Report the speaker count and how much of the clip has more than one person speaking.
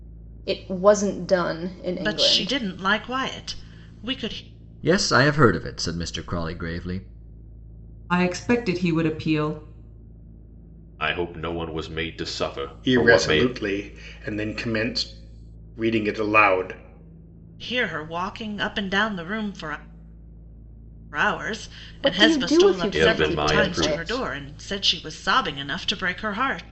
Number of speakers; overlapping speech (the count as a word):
six, about 13%